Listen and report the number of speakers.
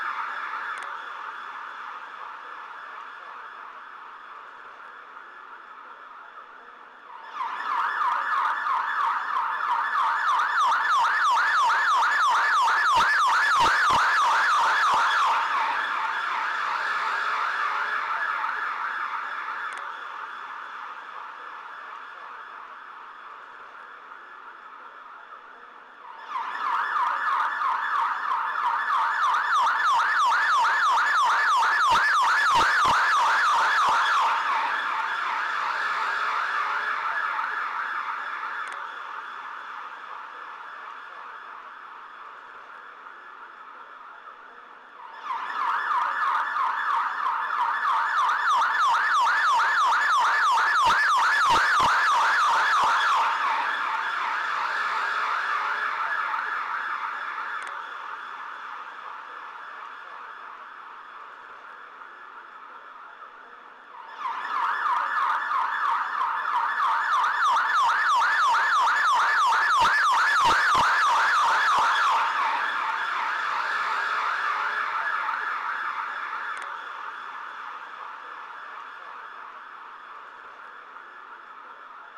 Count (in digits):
0